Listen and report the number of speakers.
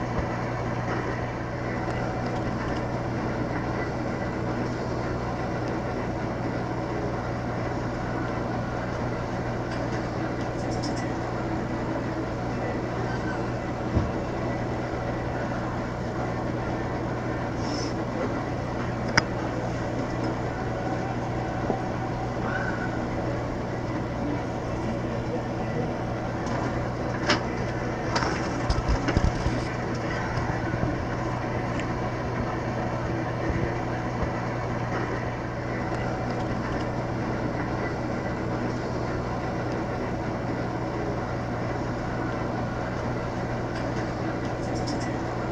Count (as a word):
zero